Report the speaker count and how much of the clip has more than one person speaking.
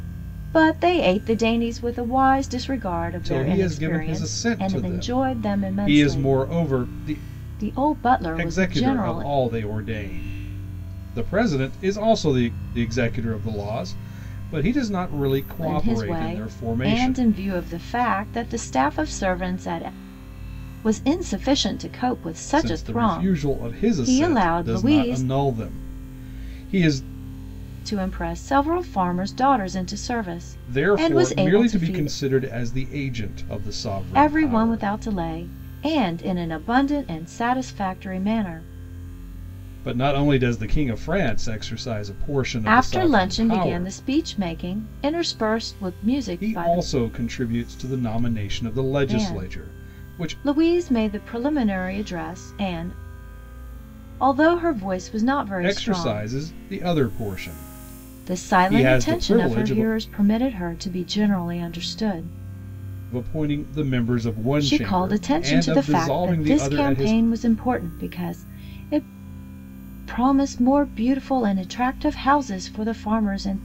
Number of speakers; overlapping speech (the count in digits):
2, about 27%